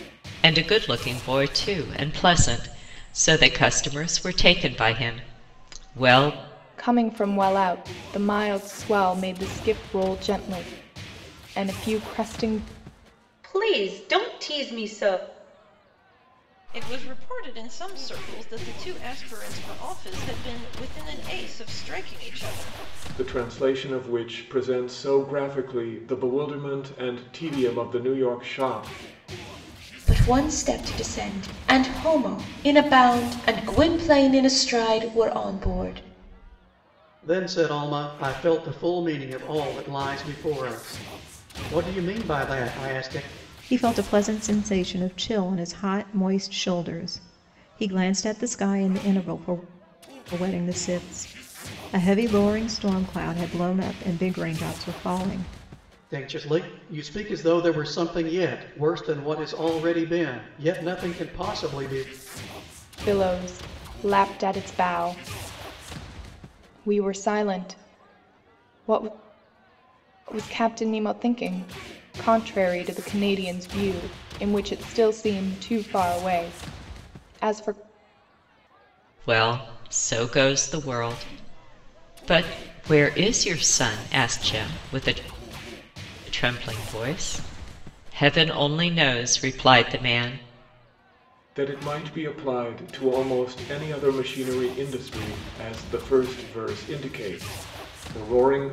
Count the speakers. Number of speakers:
eight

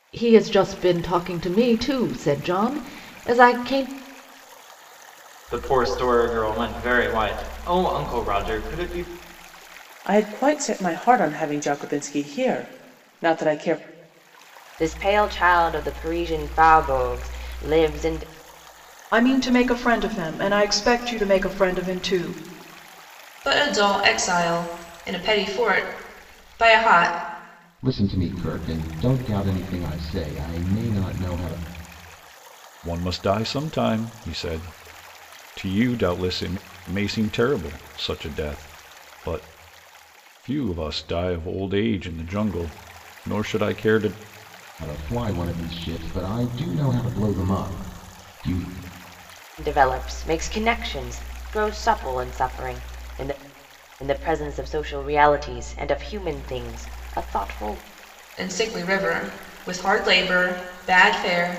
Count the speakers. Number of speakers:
eight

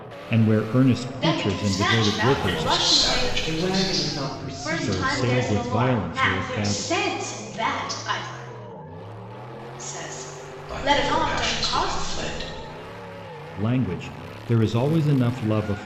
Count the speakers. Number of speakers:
four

